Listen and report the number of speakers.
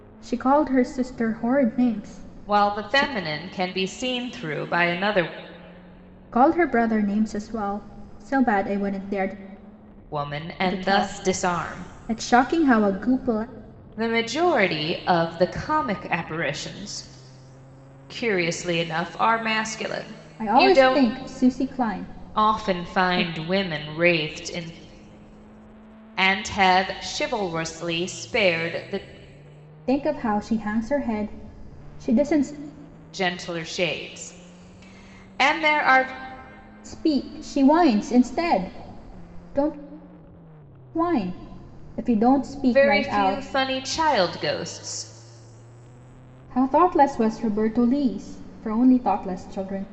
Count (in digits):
2